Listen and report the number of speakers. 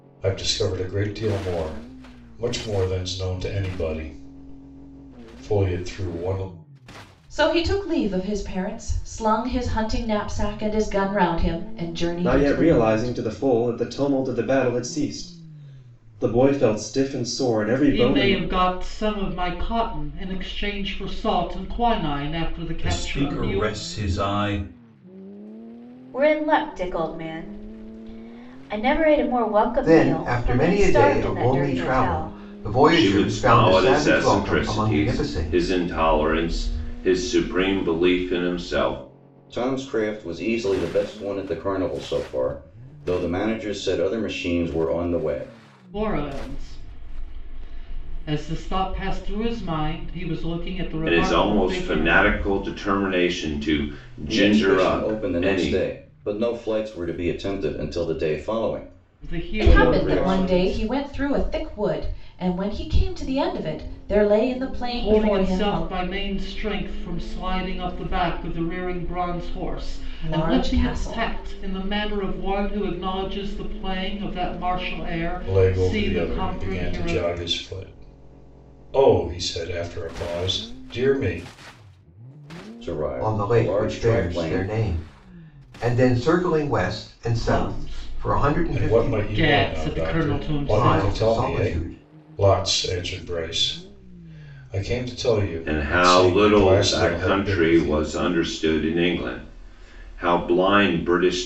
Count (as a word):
nine